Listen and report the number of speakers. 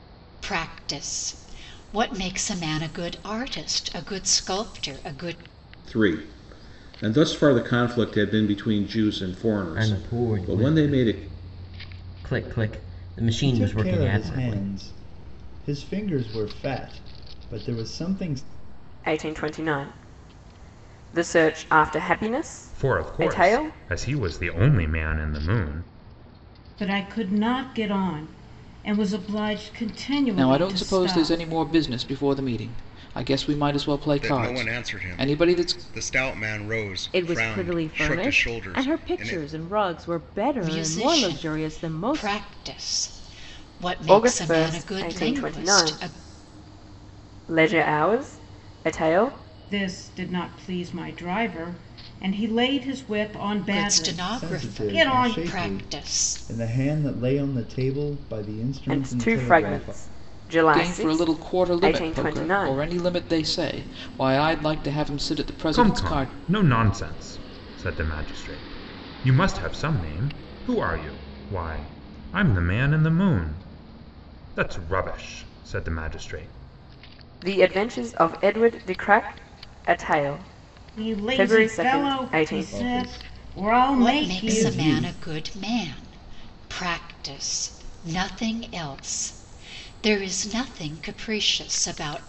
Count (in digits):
10